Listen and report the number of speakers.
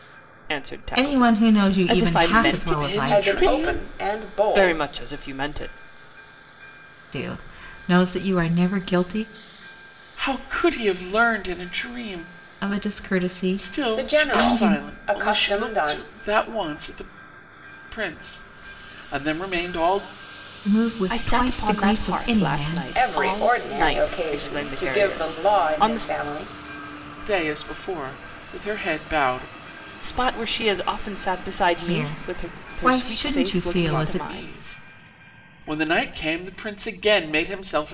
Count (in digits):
4